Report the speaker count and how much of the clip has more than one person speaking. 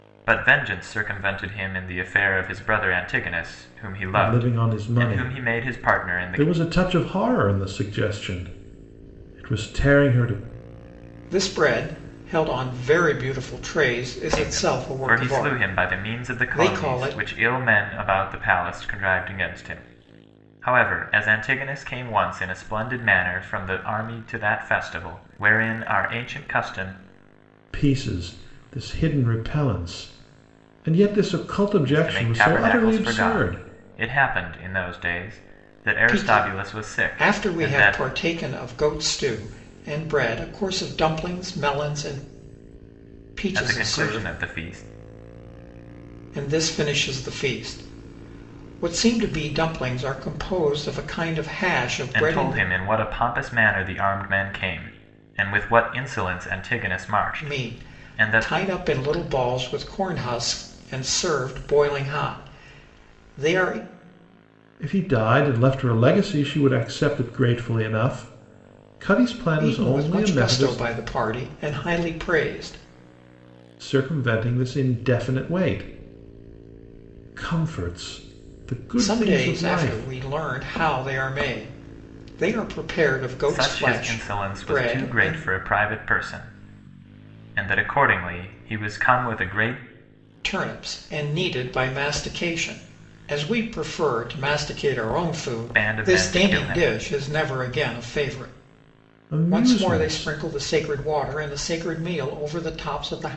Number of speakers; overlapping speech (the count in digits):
3, about 18%